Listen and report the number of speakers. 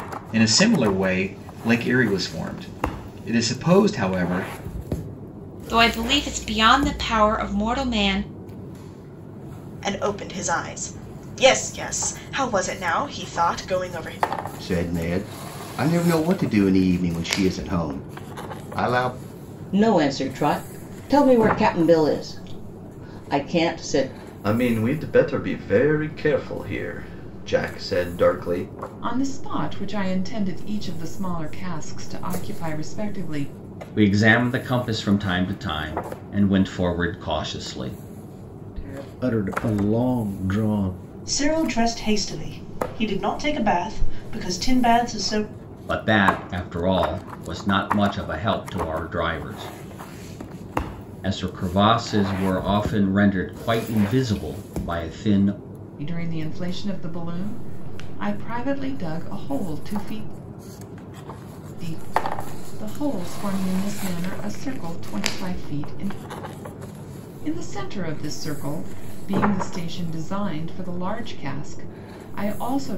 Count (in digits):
10